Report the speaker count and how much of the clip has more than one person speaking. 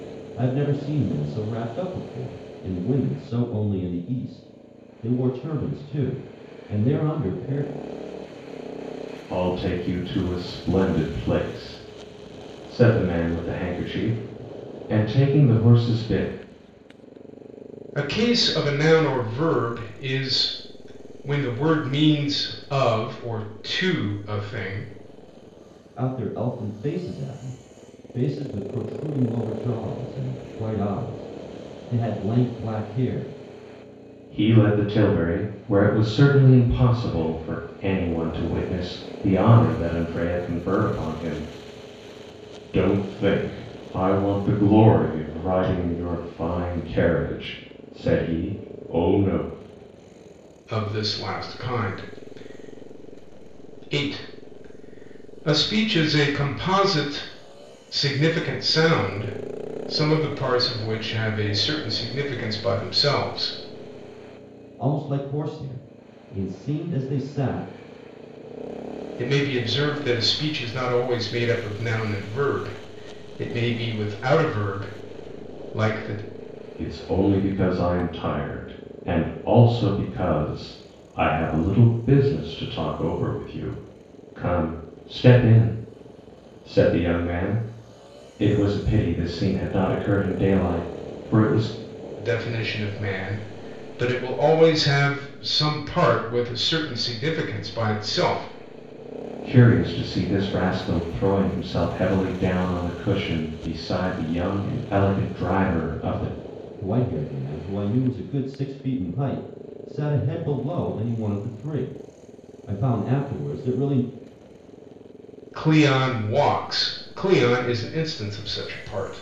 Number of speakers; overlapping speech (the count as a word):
three, no overlap